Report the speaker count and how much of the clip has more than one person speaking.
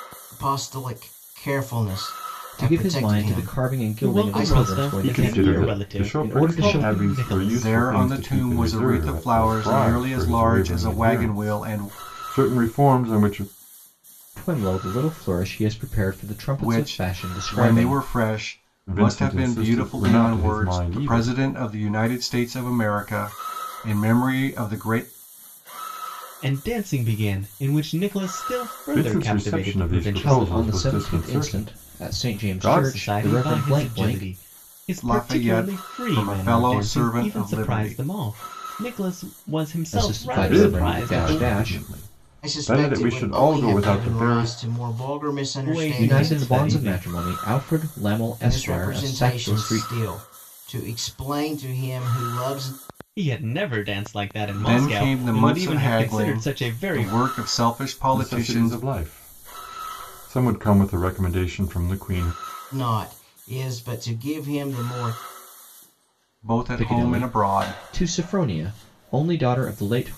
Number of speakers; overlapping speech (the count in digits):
5, about 47%